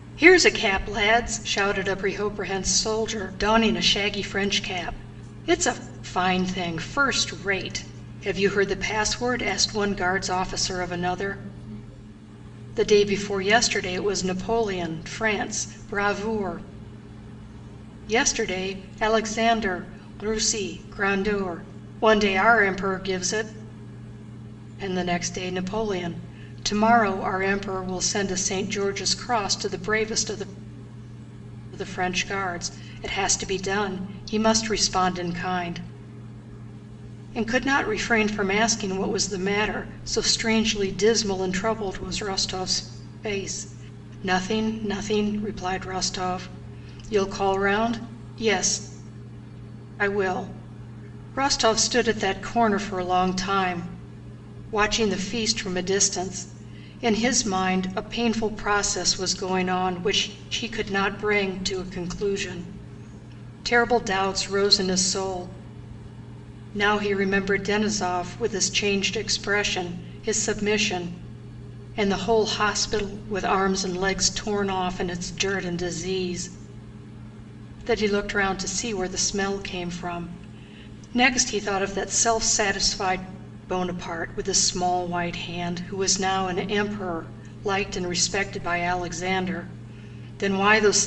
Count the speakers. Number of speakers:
1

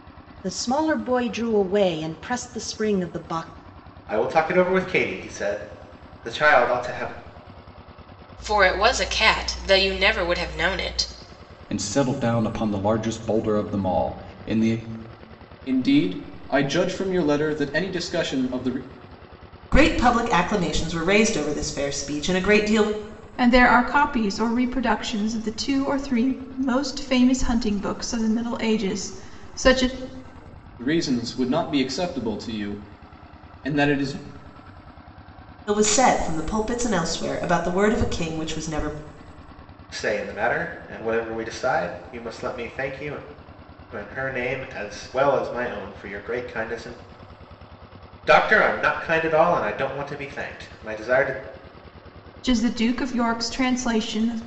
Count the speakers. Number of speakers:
7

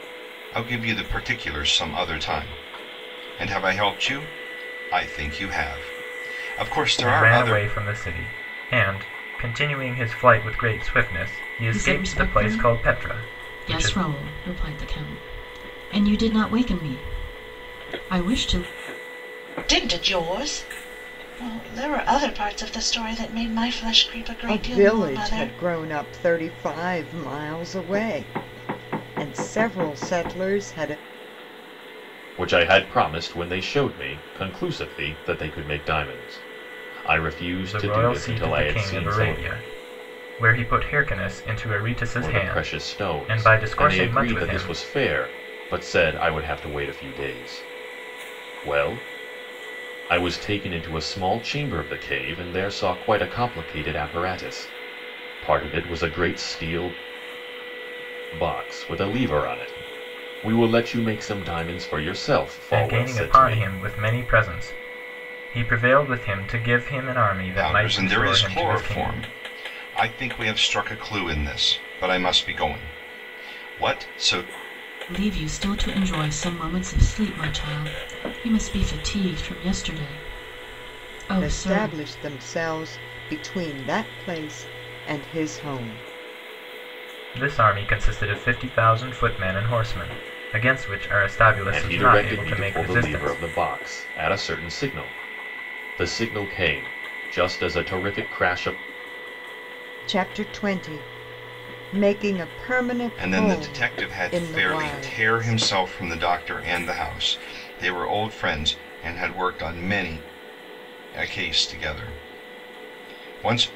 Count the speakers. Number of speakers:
6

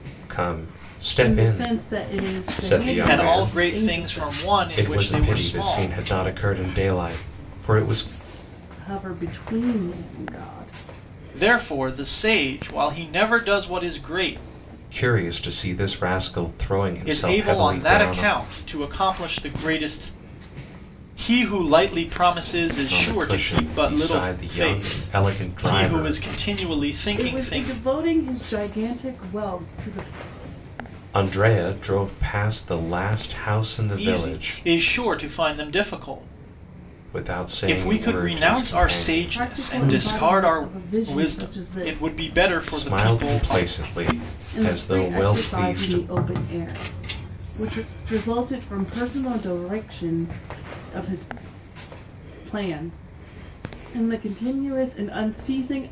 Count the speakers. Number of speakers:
3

